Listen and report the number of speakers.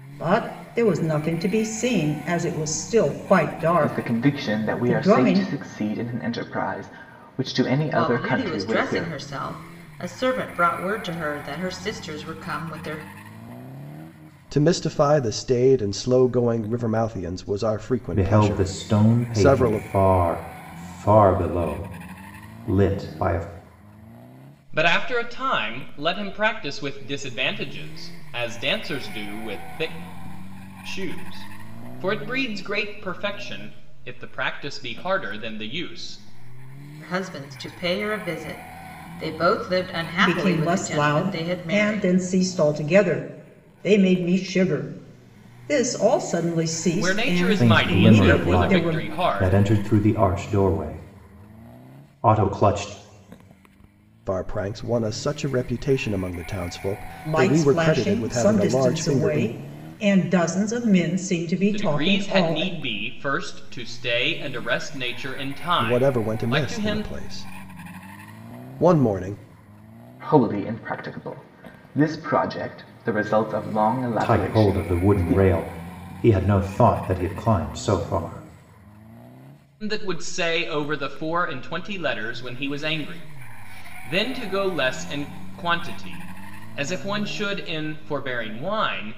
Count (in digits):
6